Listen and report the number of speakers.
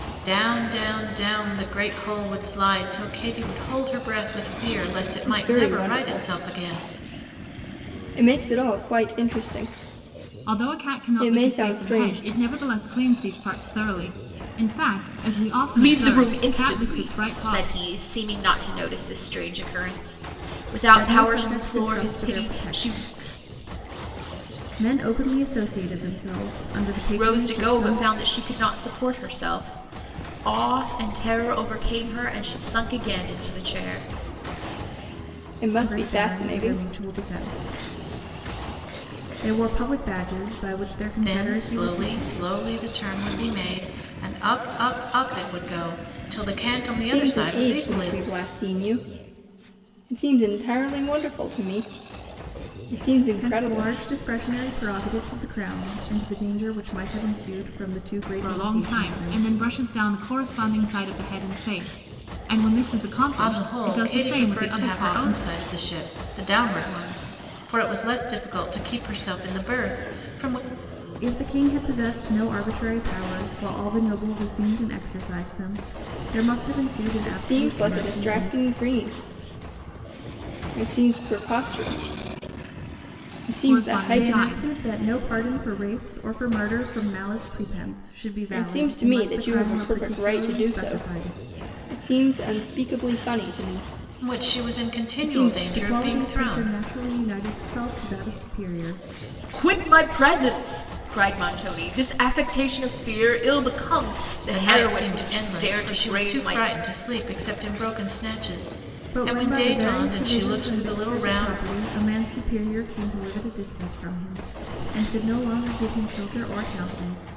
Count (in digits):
5